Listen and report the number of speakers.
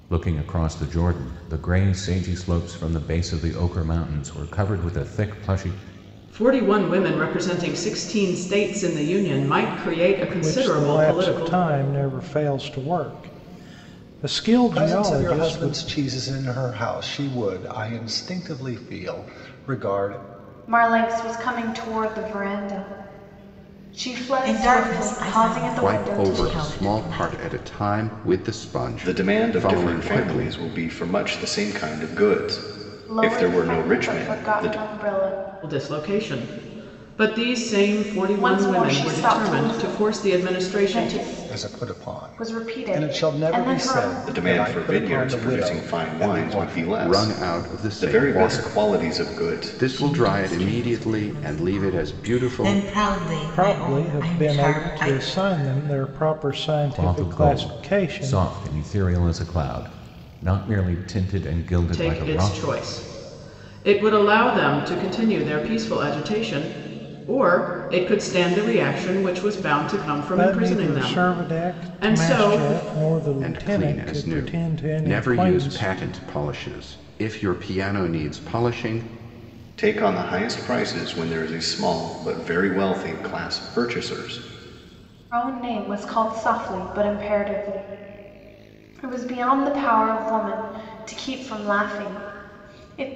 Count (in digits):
8